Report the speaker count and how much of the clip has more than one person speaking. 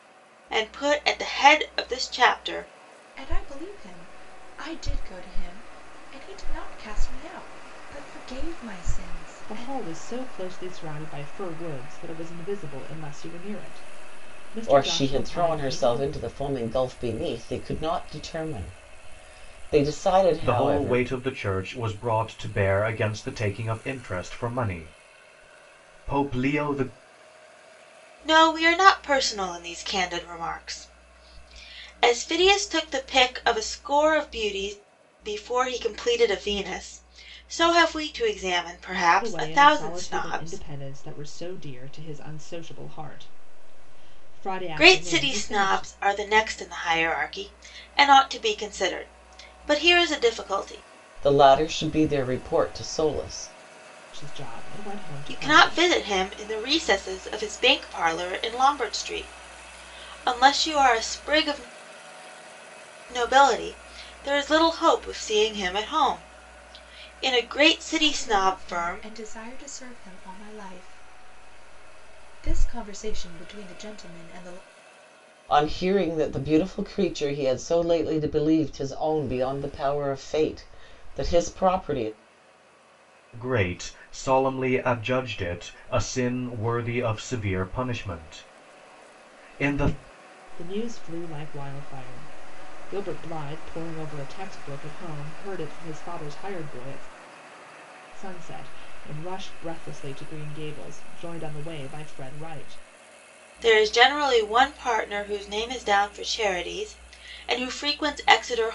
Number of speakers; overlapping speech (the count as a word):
five, about 6%